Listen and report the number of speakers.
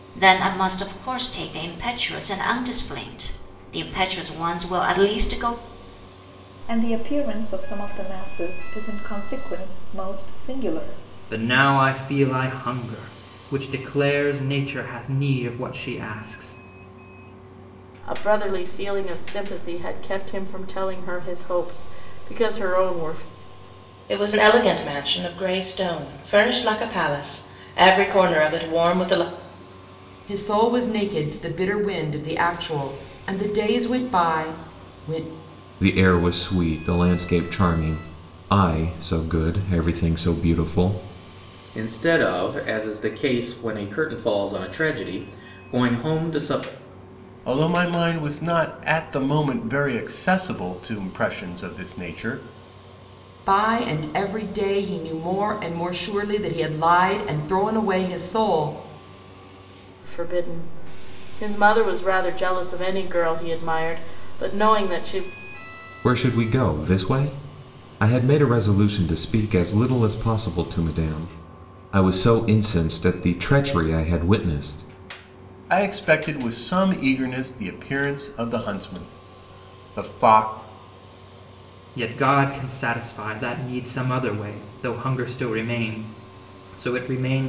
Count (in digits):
9